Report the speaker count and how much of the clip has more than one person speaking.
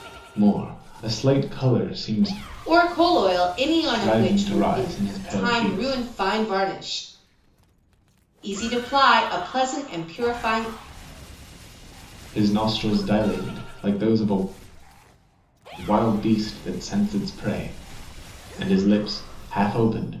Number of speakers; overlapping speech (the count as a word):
two, about 9%